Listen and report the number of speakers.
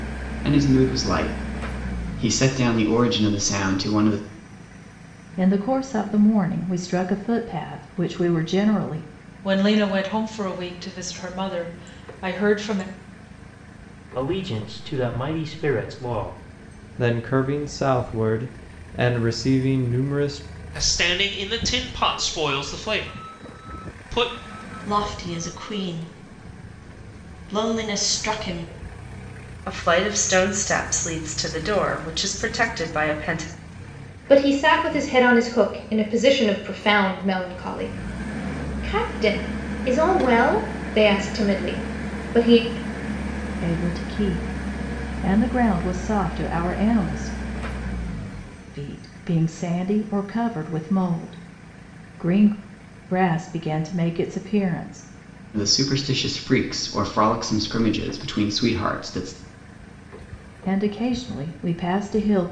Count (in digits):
9